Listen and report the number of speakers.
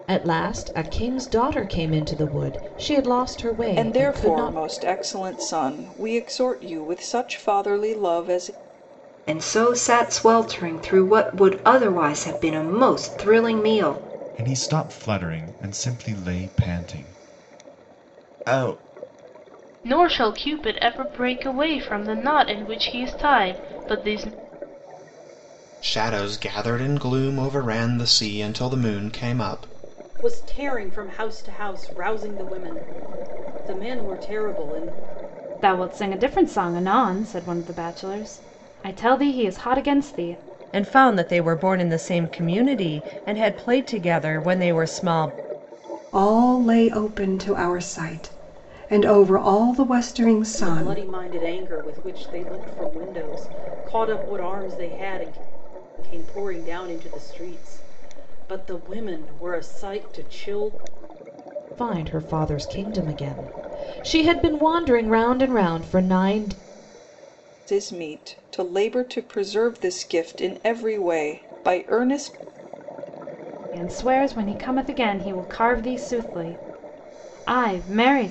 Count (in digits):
10